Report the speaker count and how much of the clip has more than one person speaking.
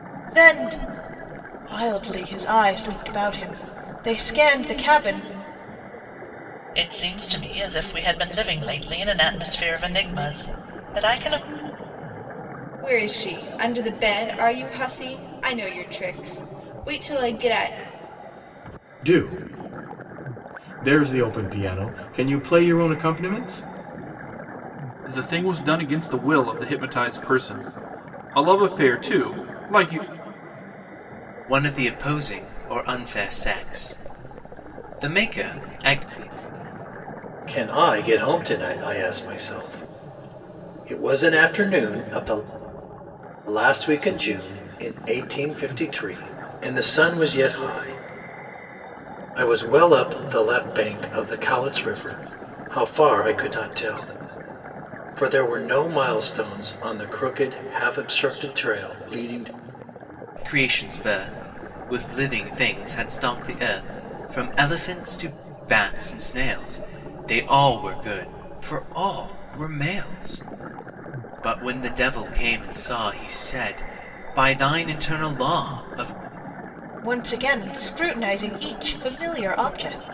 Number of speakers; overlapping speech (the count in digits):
7, no overlap